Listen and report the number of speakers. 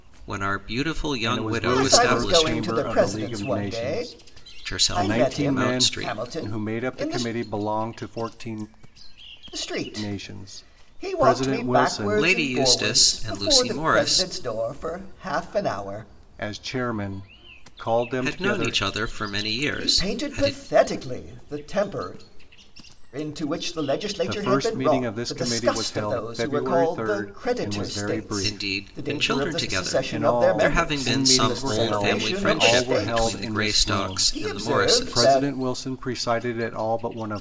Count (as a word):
three